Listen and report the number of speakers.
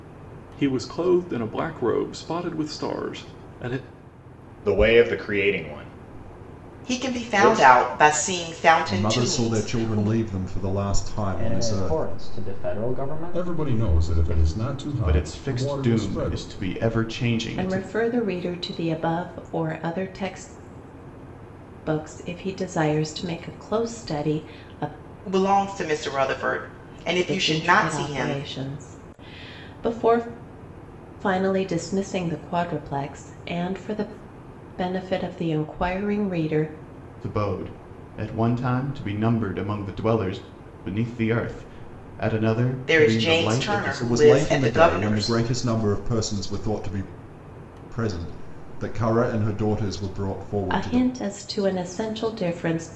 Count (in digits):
8